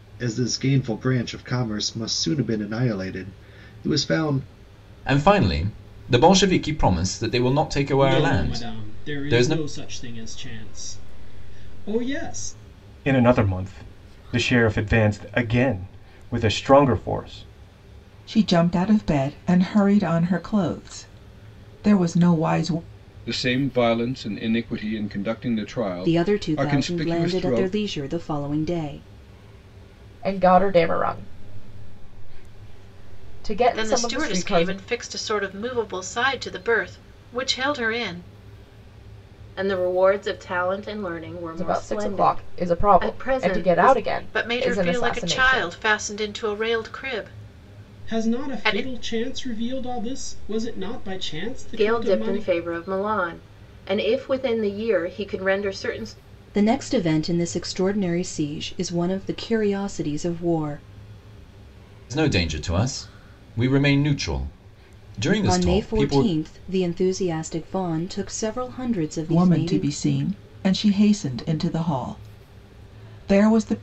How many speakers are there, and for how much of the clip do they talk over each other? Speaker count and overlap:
10, about 16%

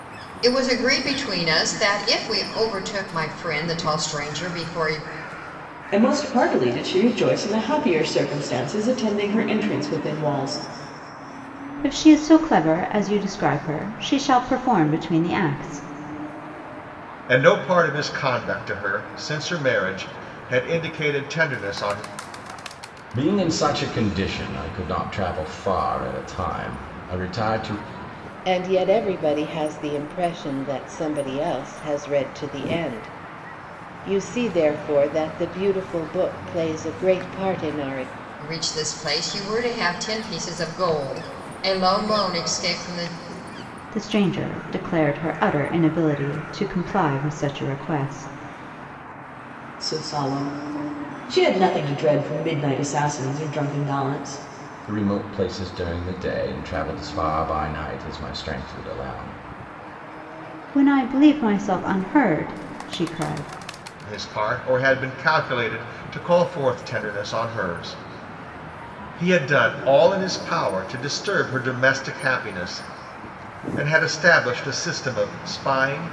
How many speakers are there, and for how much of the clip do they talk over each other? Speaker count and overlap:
6, no overlap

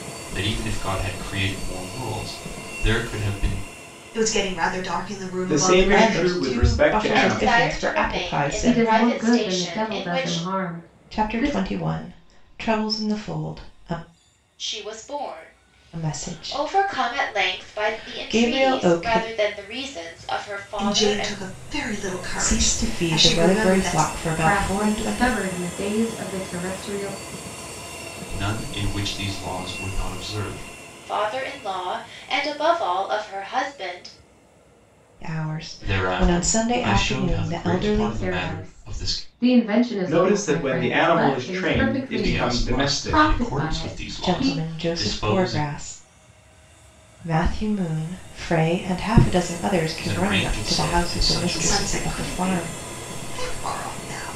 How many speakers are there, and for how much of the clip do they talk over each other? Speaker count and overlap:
6, about 44%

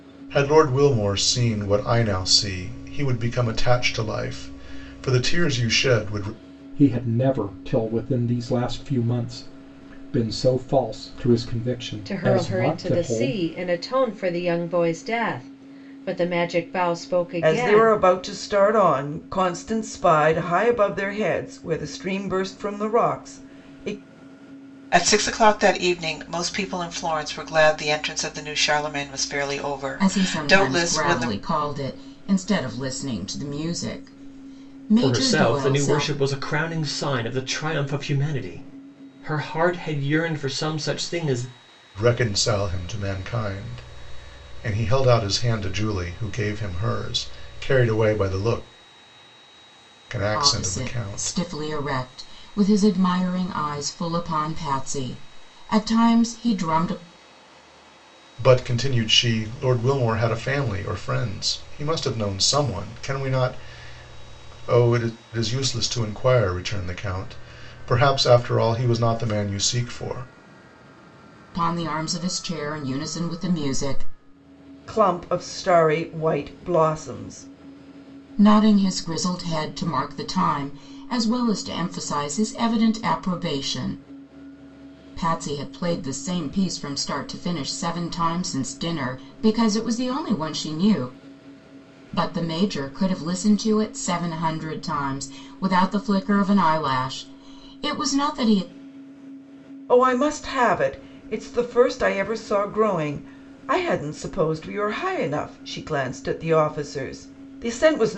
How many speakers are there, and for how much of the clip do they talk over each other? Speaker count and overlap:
7, about 5%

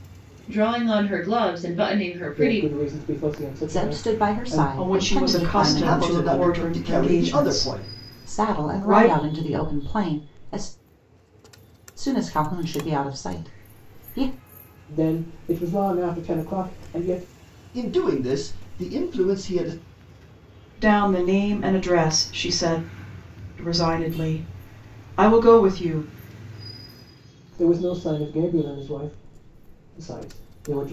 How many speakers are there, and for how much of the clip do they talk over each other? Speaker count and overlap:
5, about 18%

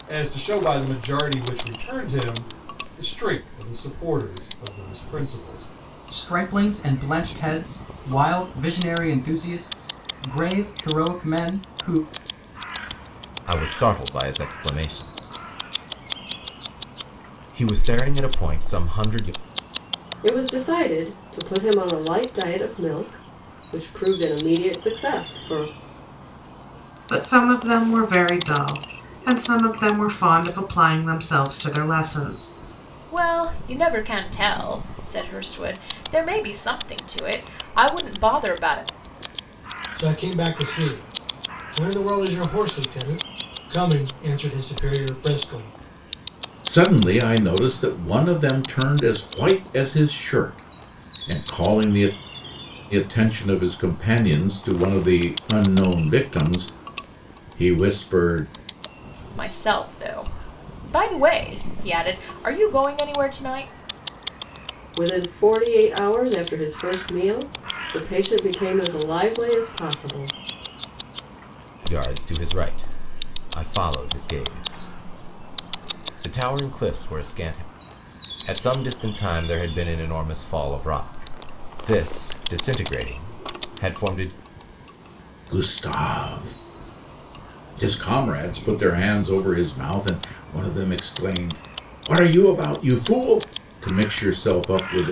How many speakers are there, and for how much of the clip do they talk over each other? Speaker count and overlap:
8, no overlap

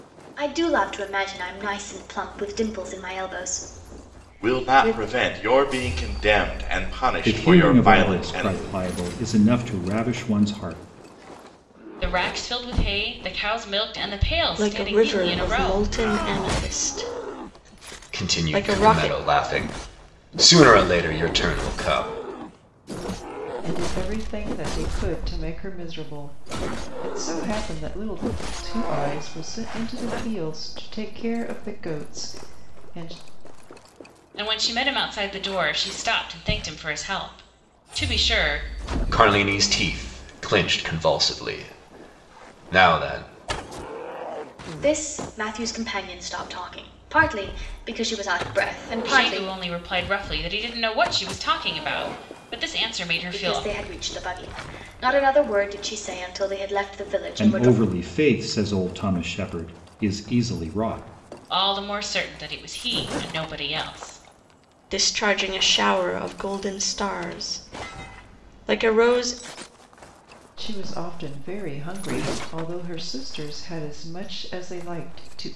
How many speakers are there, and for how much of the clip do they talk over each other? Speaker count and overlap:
7, about 8%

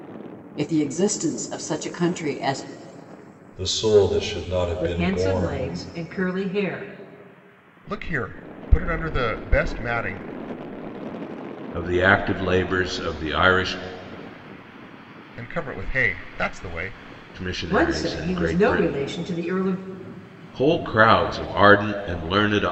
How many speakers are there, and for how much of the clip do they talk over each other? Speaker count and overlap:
5, about 10%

